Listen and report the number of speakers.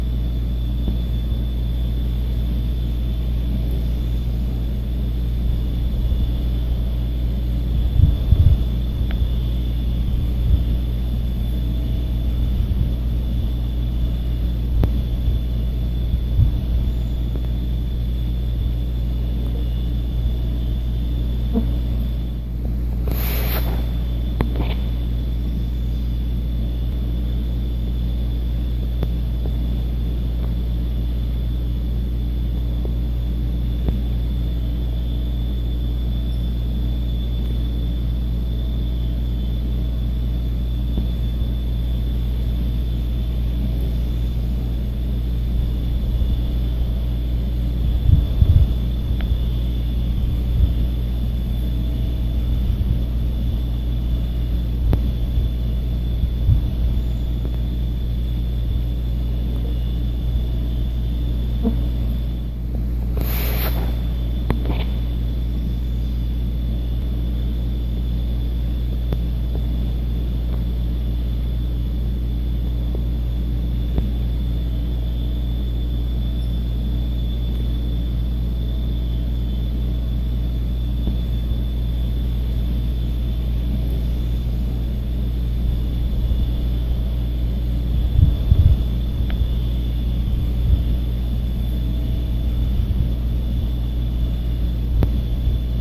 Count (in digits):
0